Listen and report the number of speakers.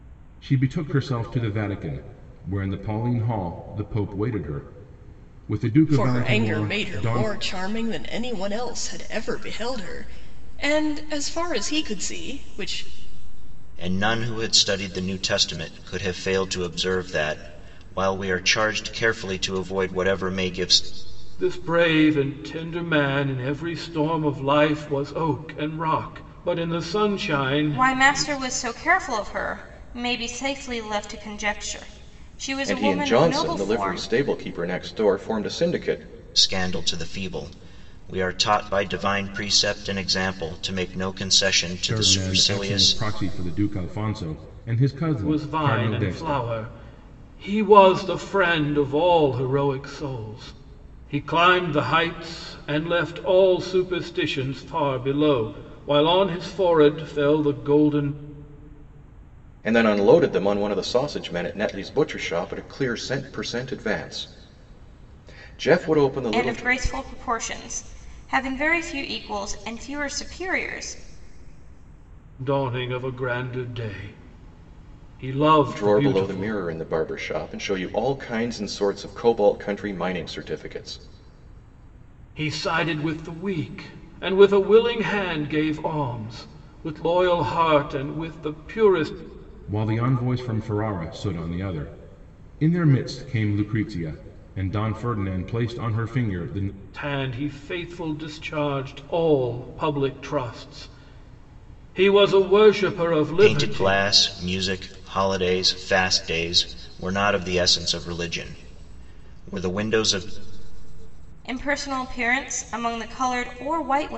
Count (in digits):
6